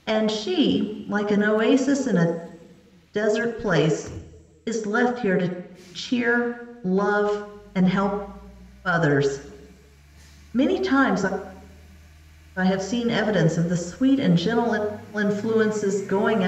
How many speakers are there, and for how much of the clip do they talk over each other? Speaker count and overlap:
one, no overlap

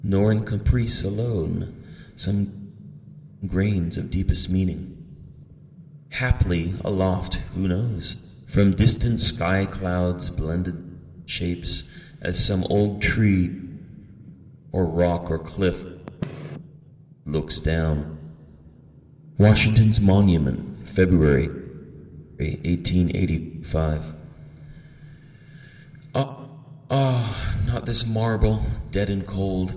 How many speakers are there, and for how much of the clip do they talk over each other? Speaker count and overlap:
one, no overlap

